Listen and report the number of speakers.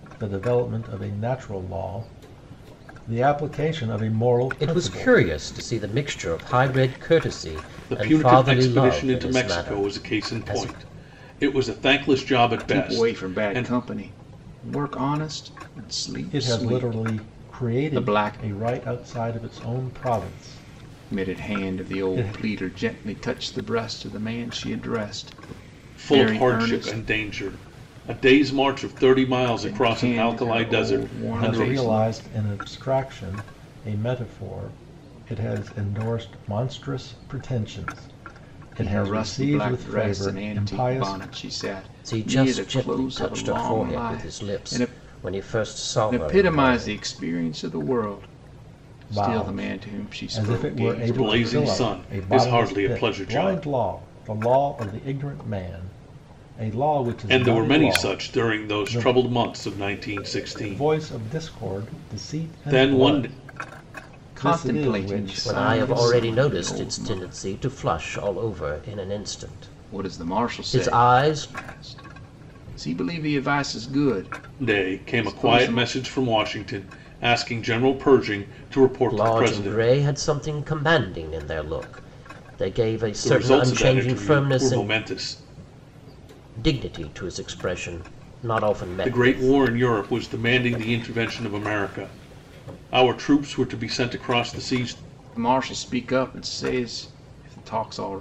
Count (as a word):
four